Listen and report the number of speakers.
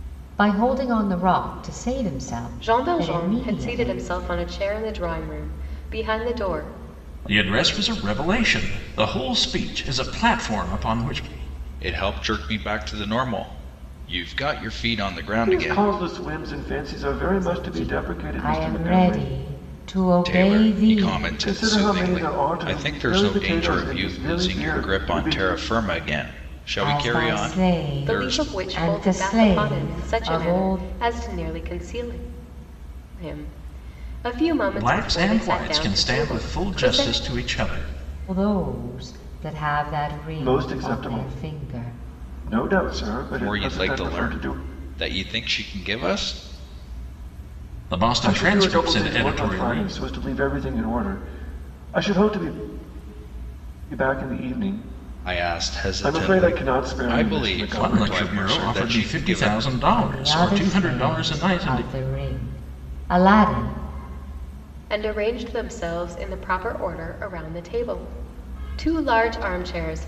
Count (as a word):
five